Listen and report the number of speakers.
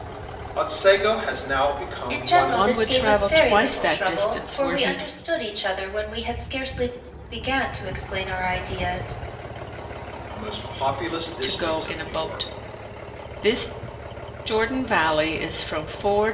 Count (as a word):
three